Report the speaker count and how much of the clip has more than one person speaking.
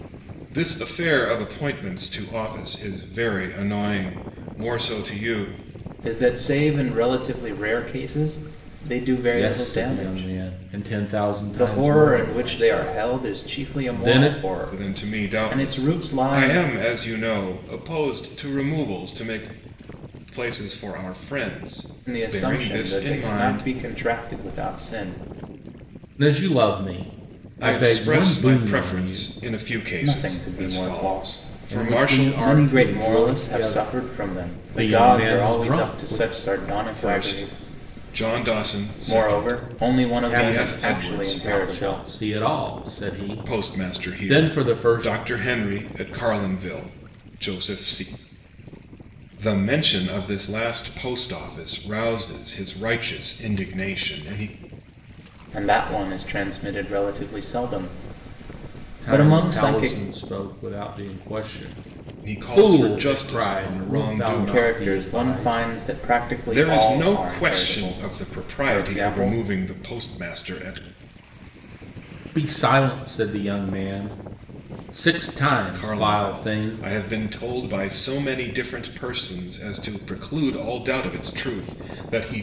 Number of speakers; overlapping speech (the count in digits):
3, about 37%